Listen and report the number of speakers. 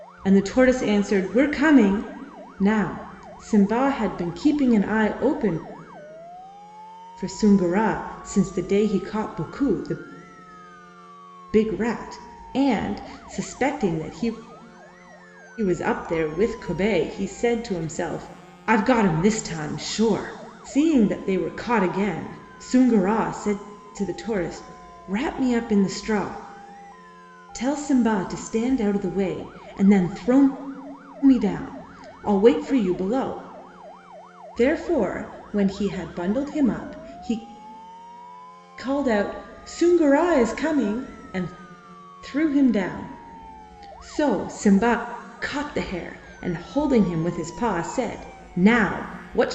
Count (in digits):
1